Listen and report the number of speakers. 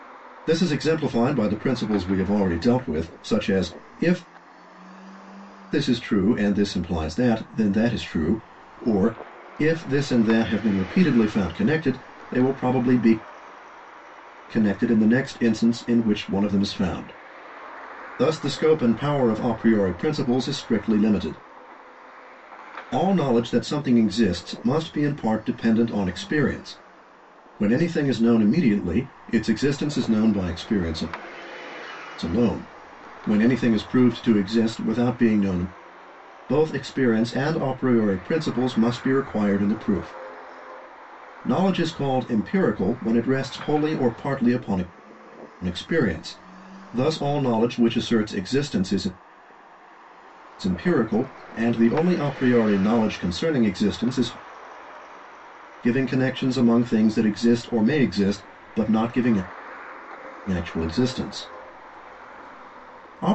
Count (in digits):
1